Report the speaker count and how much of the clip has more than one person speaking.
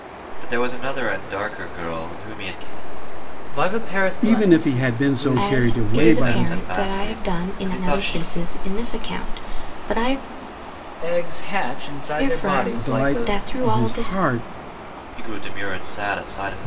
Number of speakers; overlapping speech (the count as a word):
four, about 36%